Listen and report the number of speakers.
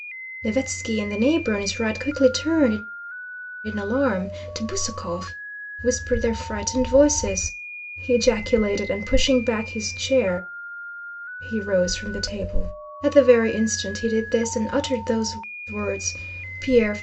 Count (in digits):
1